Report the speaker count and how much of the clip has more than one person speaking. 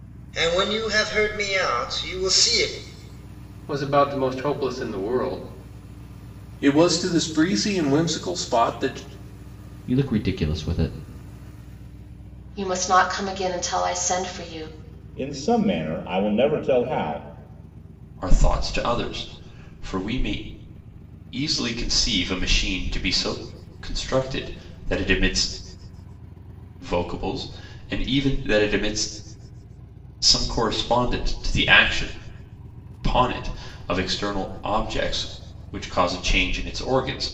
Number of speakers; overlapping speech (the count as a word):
seven, no overlap